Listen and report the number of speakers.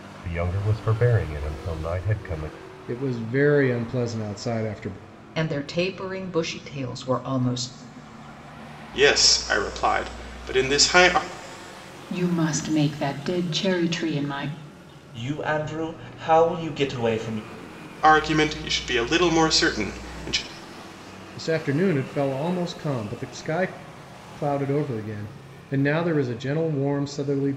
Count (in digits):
6